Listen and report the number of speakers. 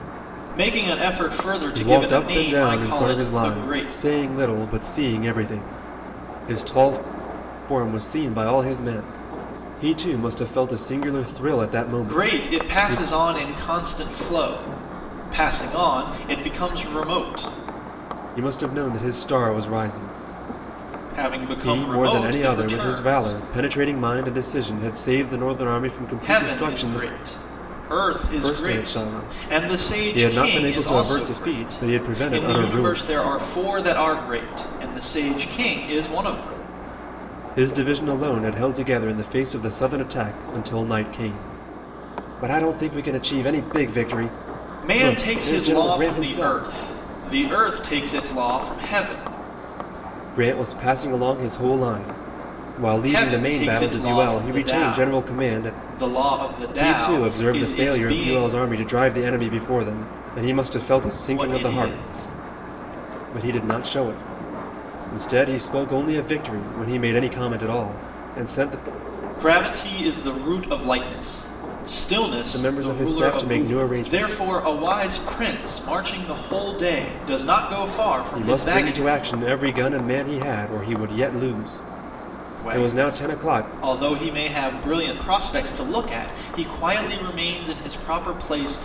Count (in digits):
2